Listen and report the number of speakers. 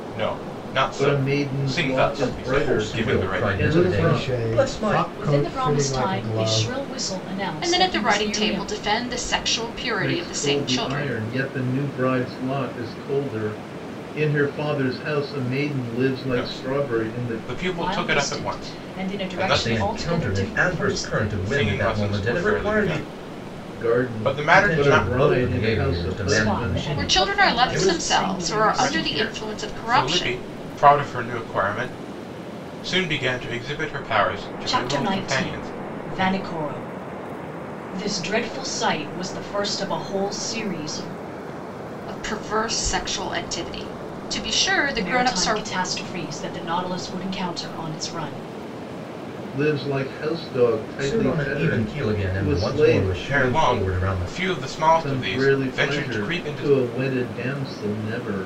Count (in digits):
6